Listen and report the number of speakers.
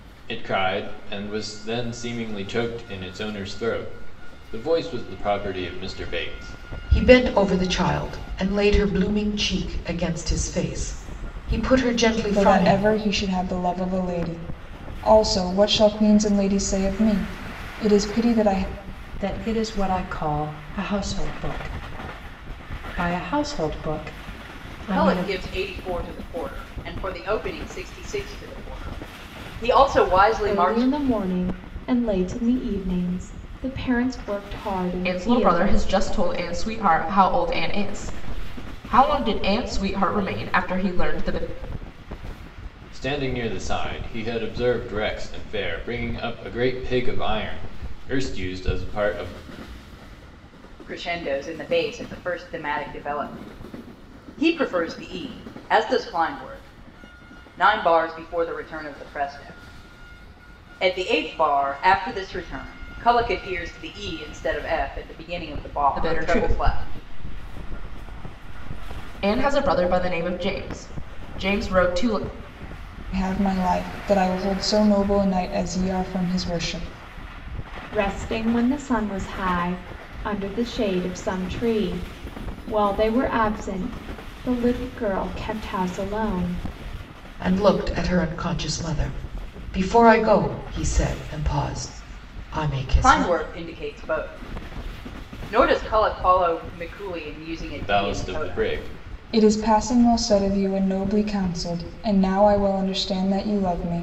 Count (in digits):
7